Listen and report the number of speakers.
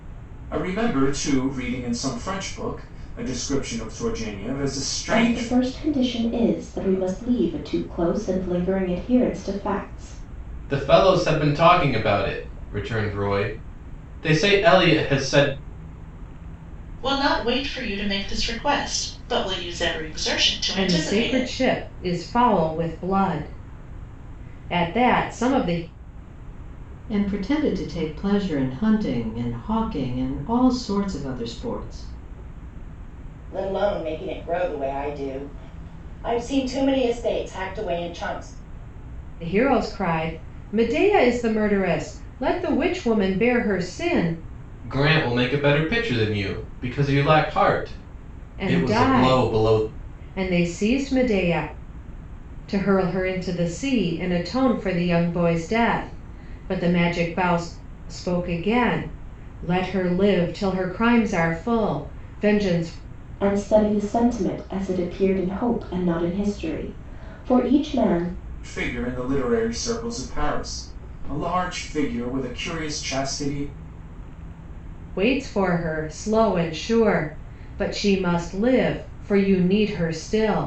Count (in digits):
7